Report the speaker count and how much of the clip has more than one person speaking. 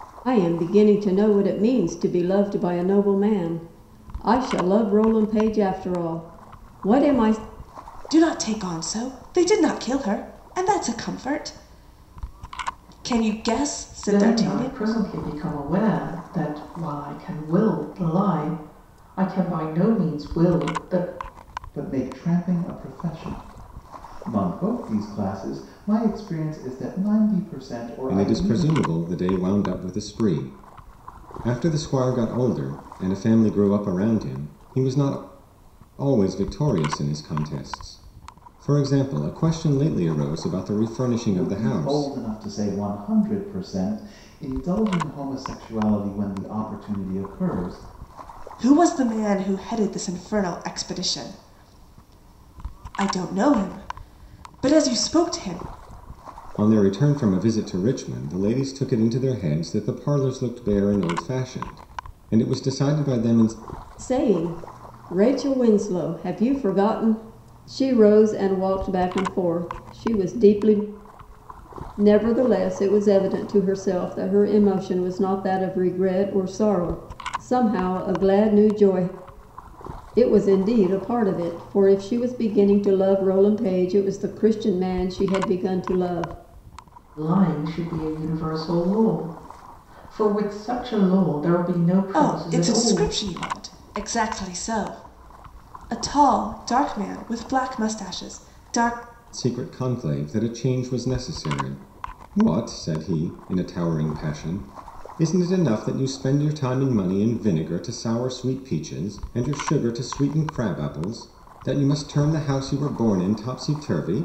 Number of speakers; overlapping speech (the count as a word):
five, about 3%